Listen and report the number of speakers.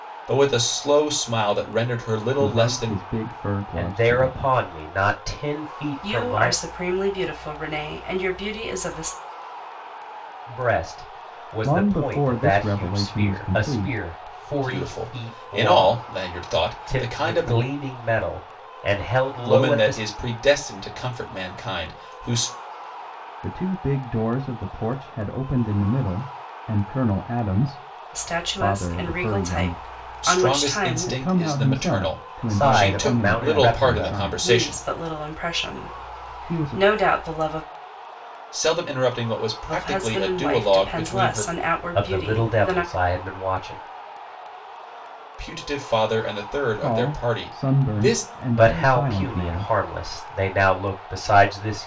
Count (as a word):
four